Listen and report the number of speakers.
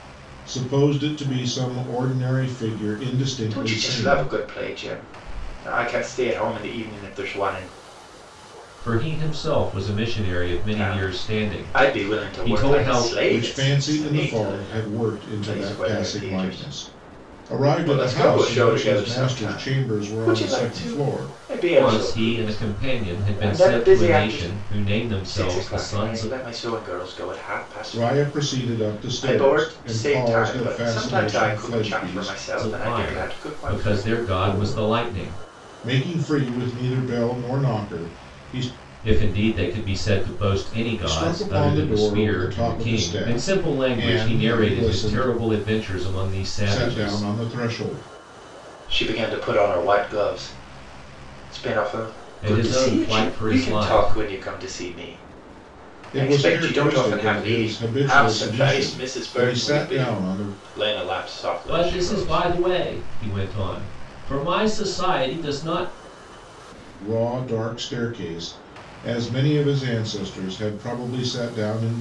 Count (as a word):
three